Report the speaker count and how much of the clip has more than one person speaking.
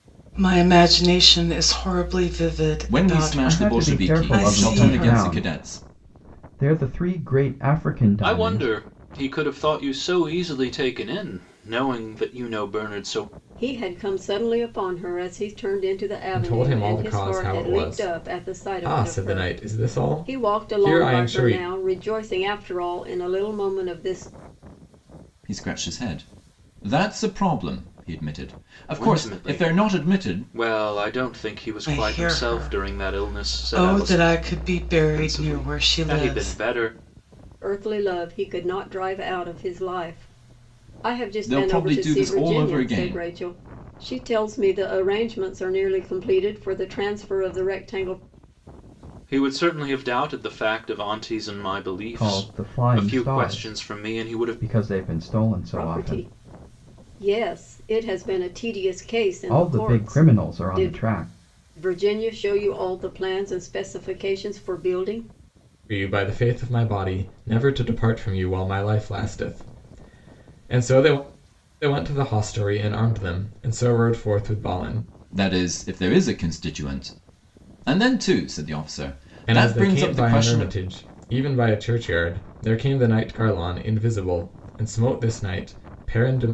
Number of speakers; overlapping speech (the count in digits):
6, about 25%